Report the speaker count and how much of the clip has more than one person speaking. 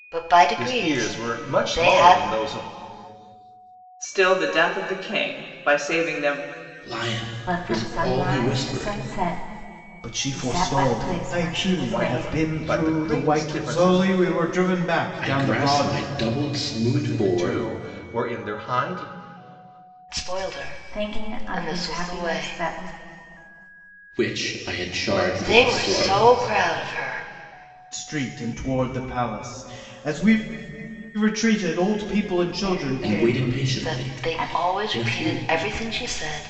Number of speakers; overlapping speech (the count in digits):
6, about 40%